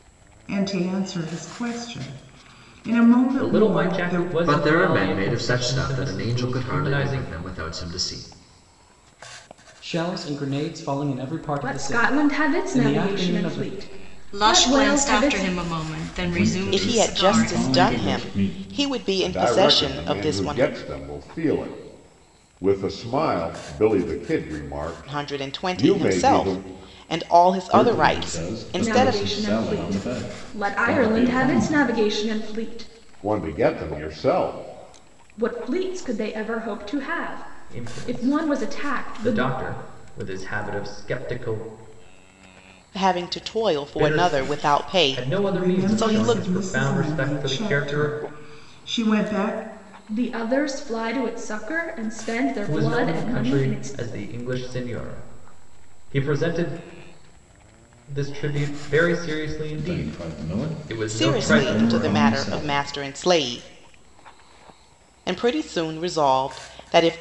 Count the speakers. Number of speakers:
nine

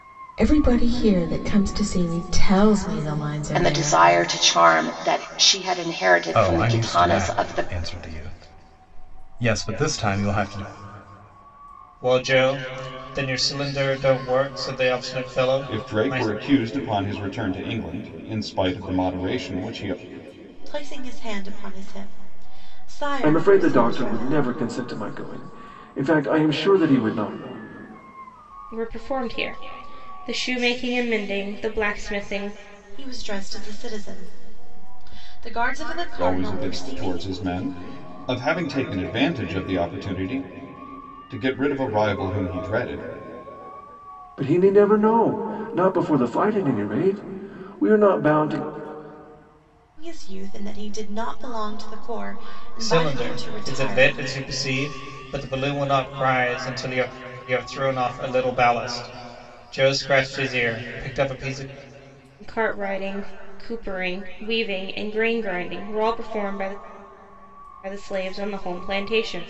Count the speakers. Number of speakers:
eight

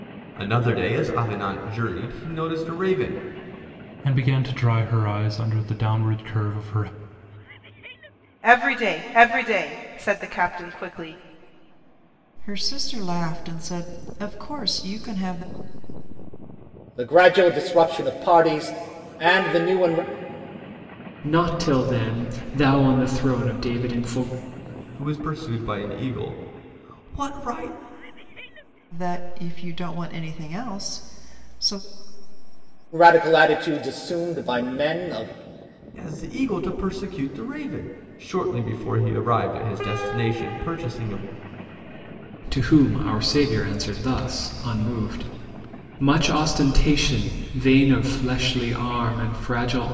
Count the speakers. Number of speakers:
six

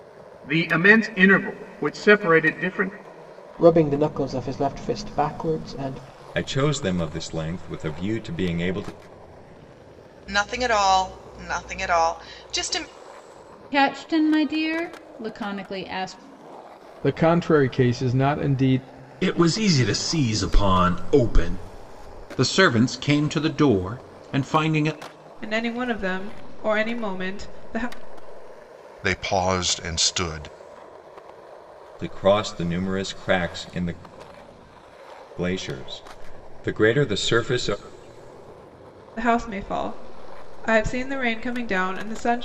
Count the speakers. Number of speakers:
ten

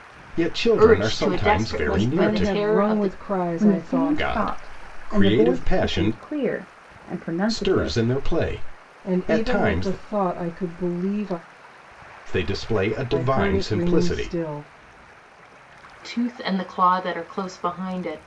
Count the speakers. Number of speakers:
four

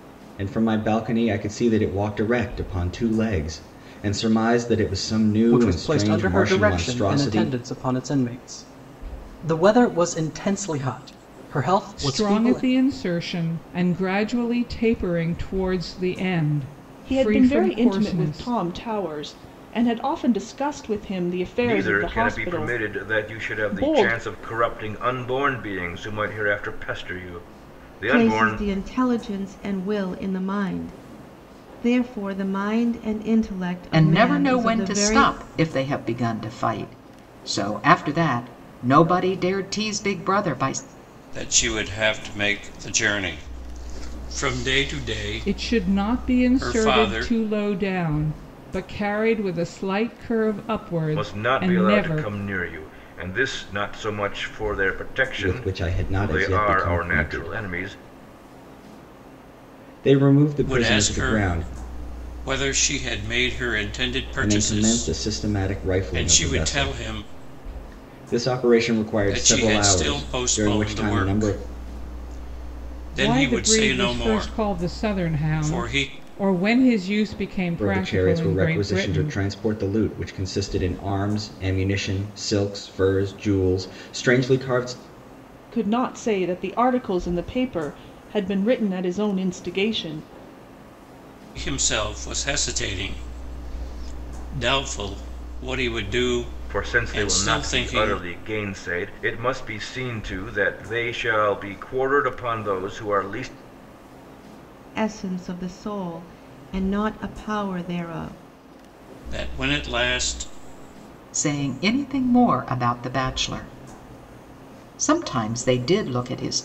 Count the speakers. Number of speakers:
eight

